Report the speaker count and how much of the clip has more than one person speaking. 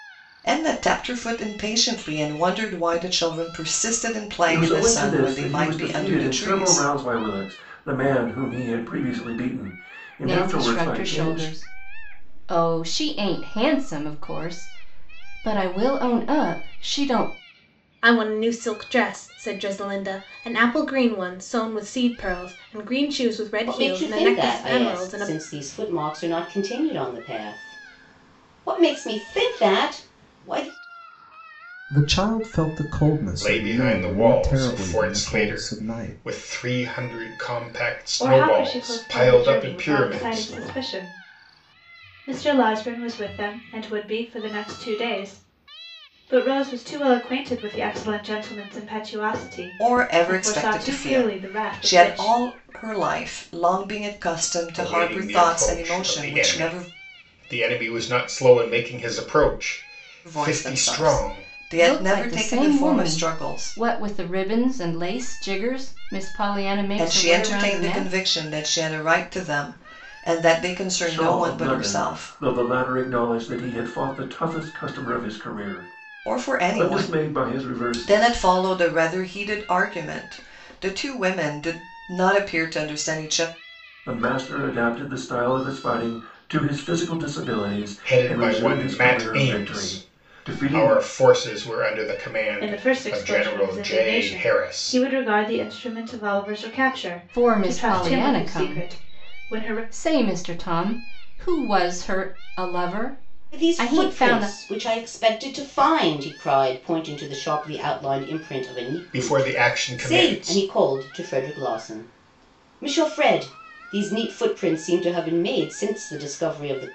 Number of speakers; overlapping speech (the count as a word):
eight, about 29%